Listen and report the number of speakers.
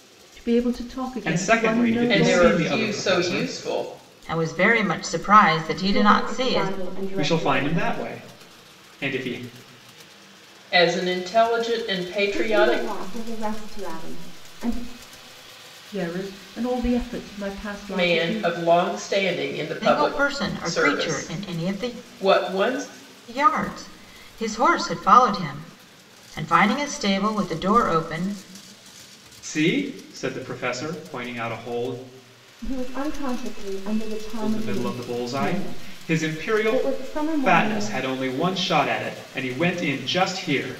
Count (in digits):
5